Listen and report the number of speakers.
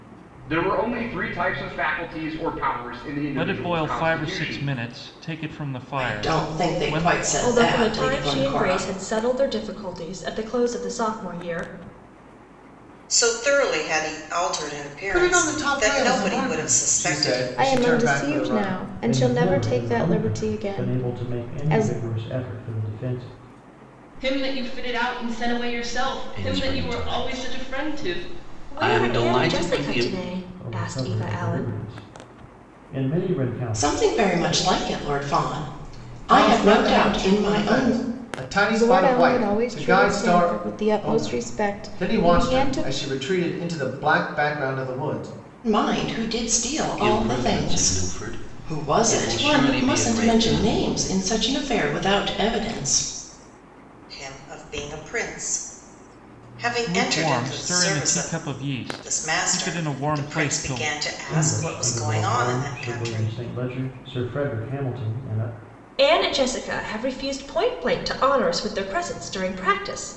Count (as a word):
ten